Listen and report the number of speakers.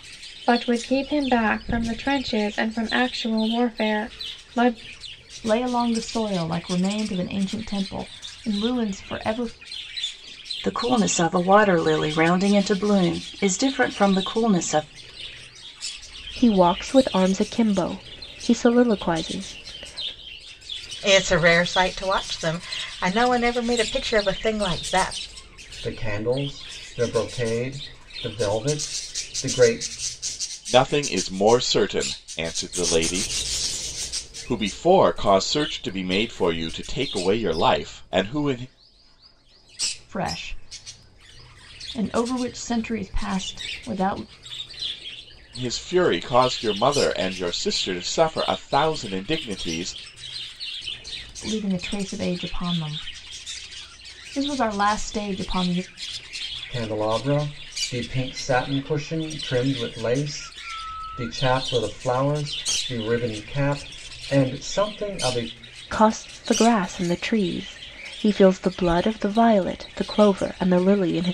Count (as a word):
seven